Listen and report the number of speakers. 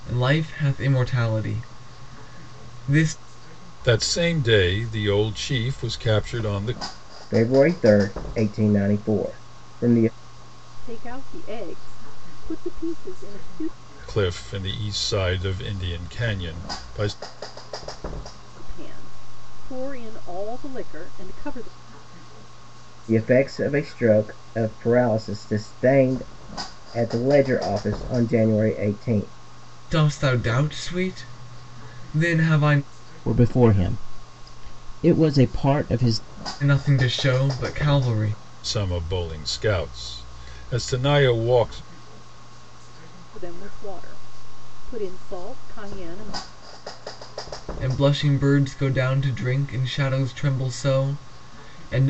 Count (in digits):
4